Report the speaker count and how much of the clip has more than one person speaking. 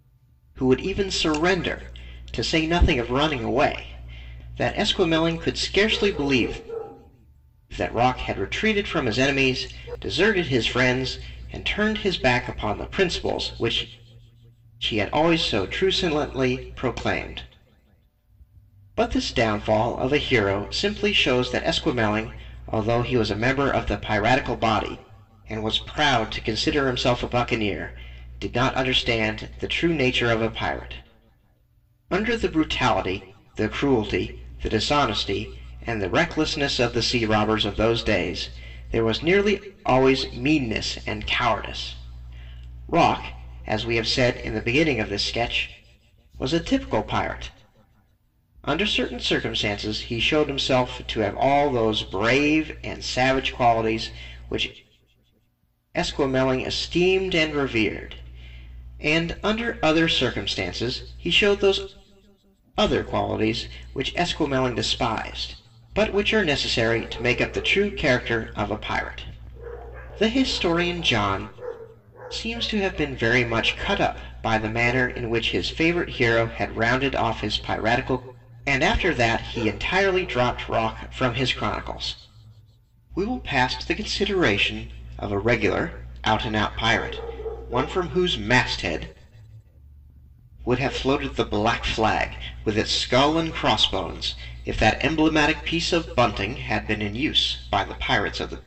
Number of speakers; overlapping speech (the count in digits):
1, no overlap